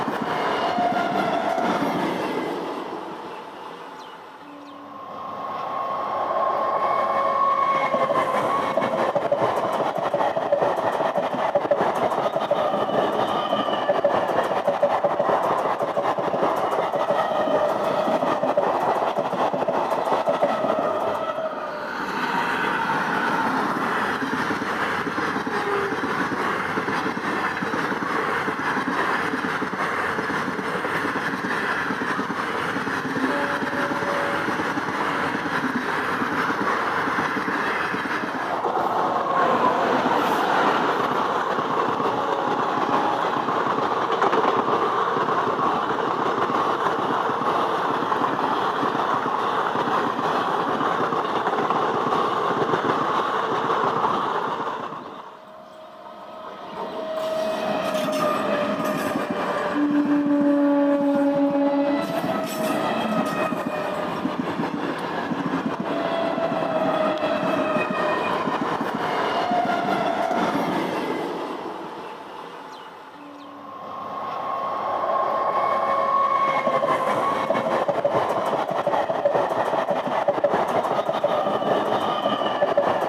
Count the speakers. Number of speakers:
zero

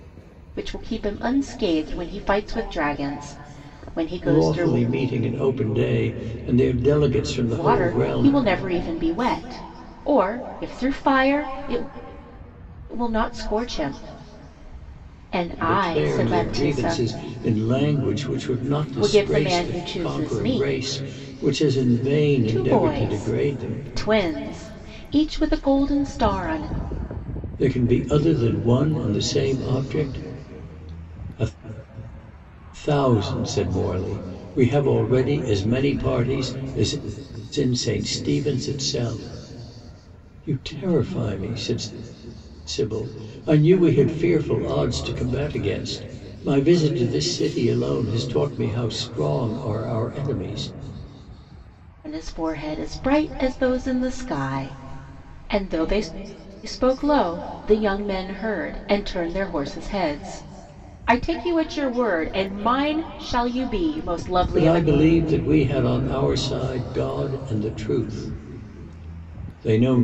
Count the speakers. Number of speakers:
two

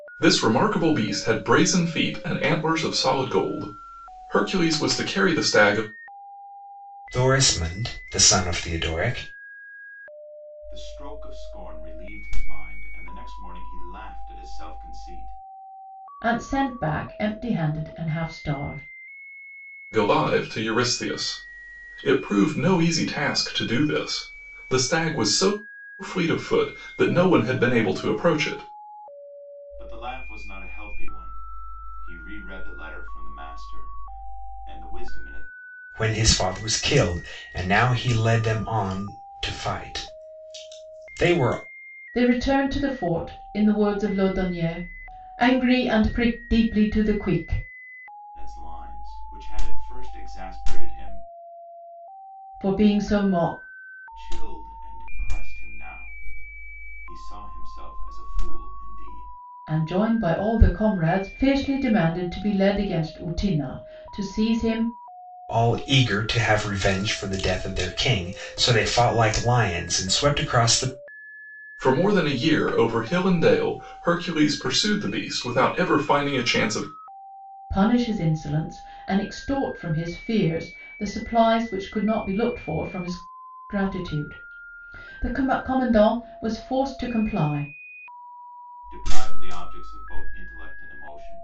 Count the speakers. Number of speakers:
four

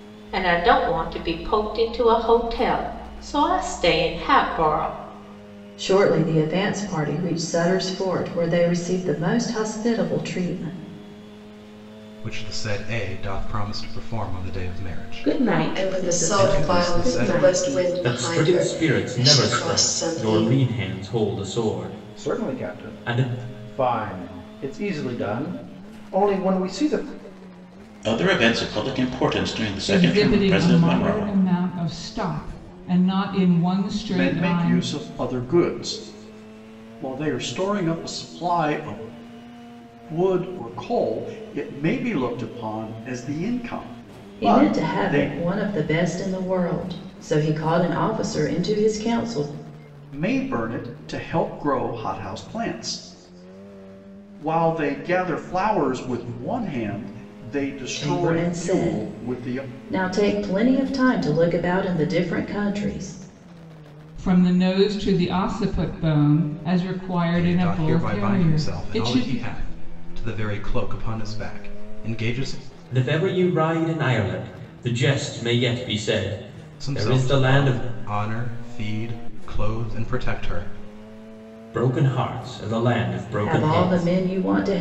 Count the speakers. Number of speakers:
ten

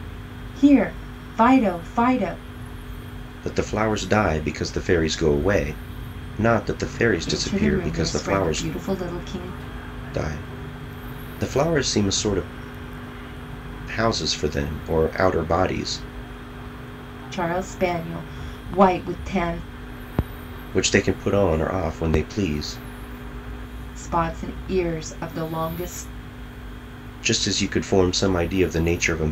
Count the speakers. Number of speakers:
two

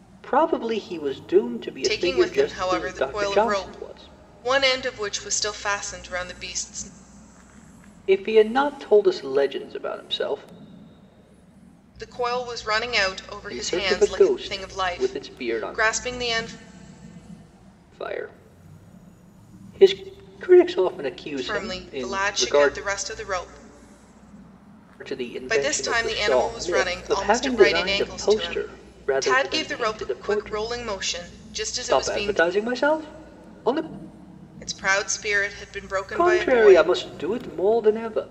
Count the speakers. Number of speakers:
two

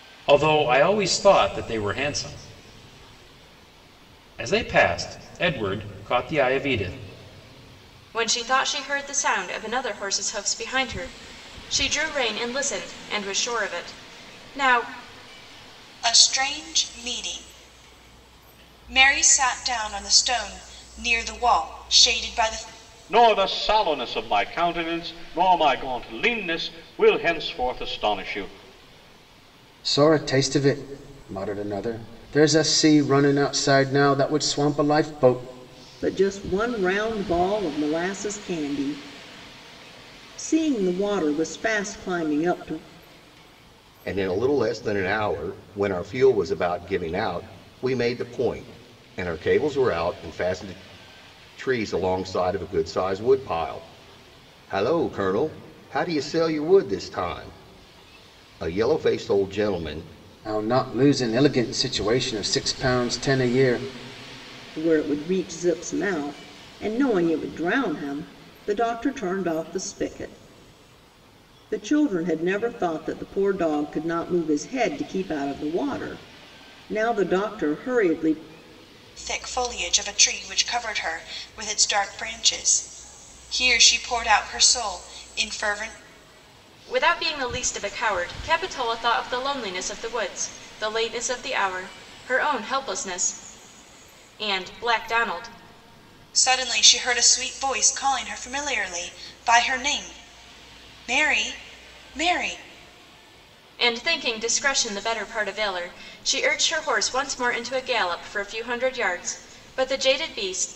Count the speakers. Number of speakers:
seven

